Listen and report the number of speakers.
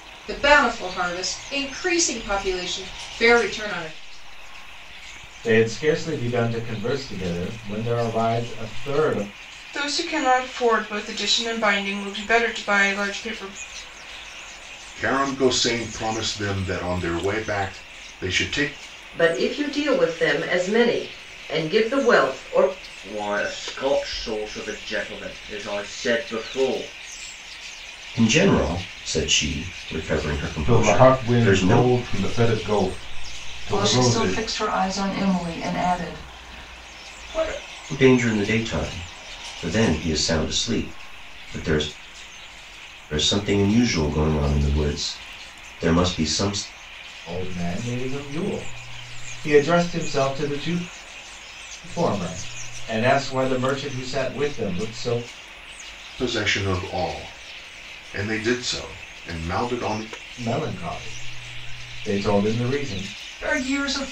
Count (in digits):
9